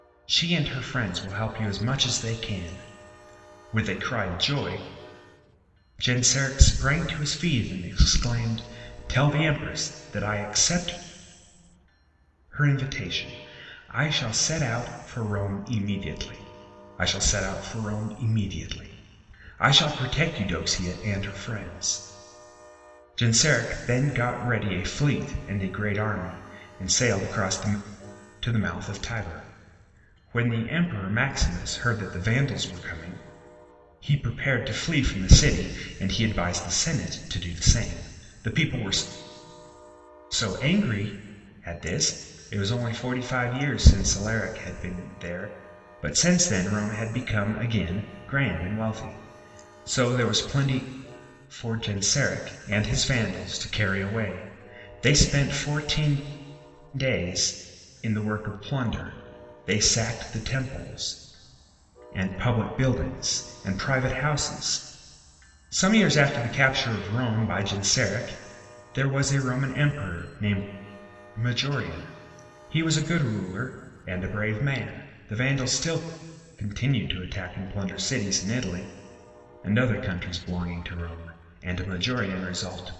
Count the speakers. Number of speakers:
1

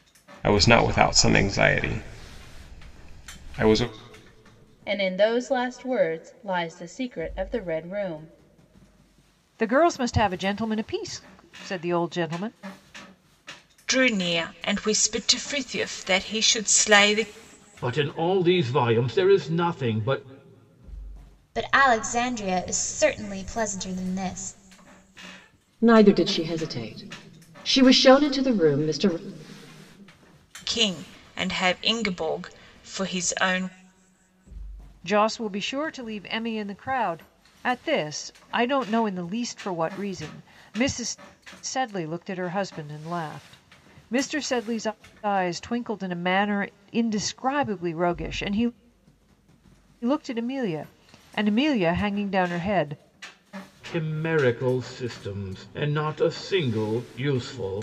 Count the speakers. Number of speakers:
7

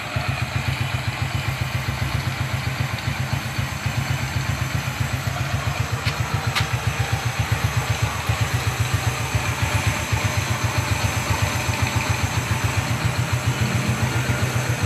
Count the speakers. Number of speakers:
0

